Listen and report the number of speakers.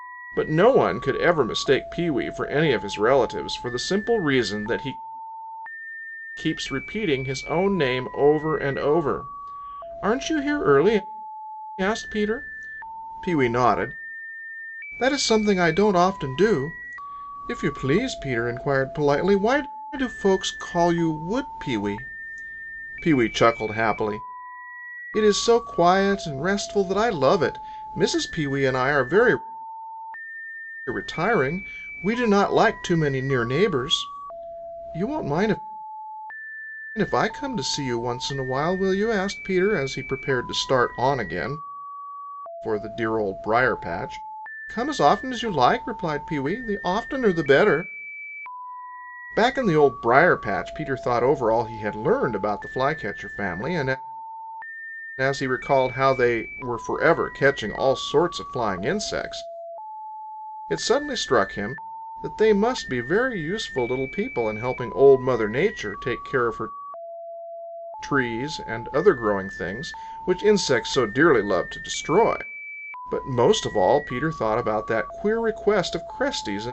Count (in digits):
1